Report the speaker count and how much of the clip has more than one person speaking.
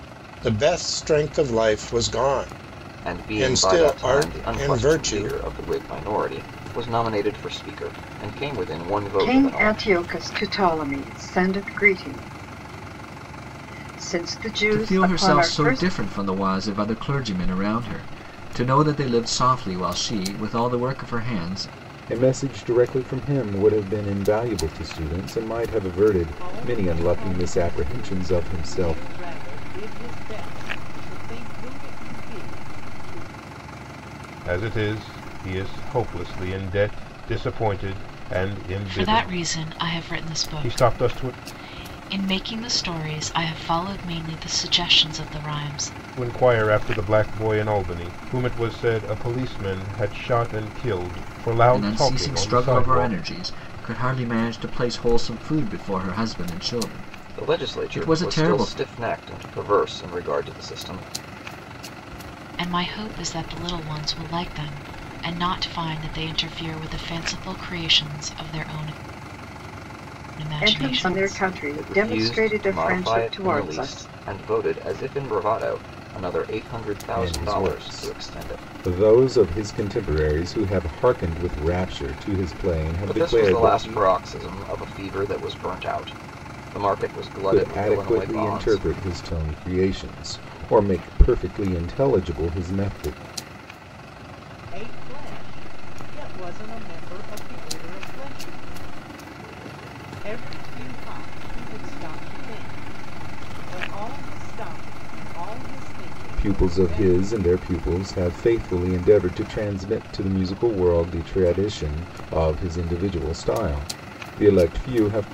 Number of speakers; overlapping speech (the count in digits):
8, about 18%